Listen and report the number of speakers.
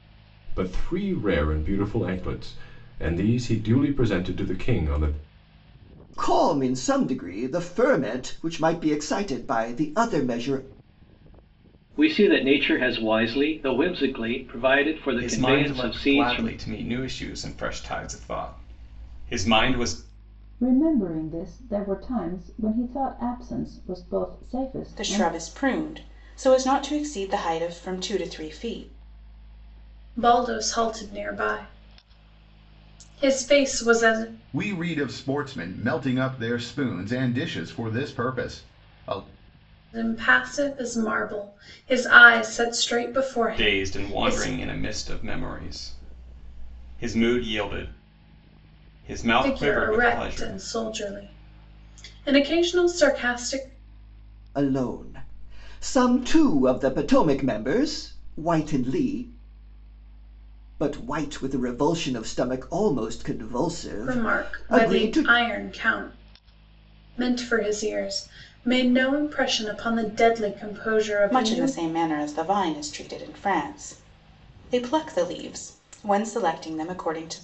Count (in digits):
8